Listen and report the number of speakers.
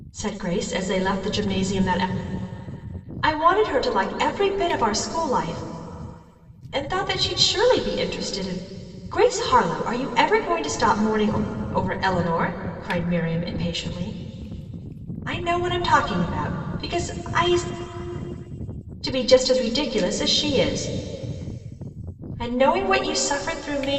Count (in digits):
1